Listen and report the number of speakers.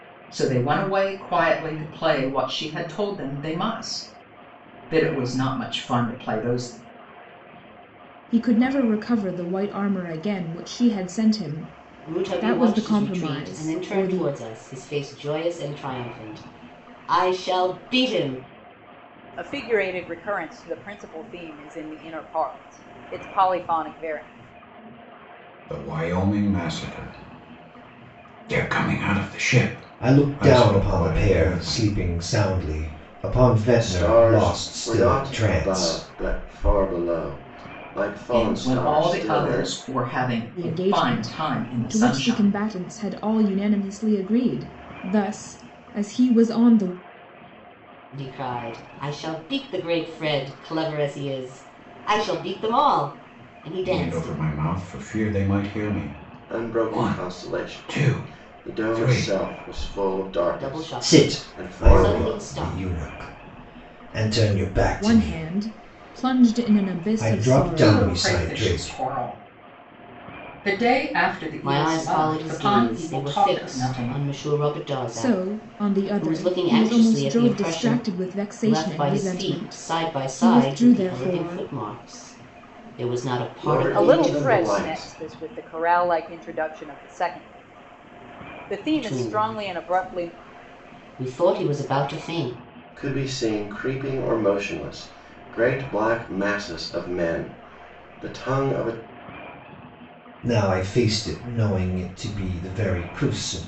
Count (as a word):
seven